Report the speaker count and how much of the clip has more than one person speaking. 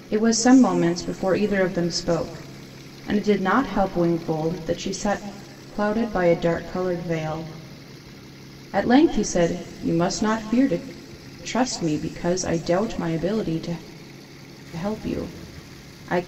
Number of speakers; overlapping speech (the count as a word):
one, no overlap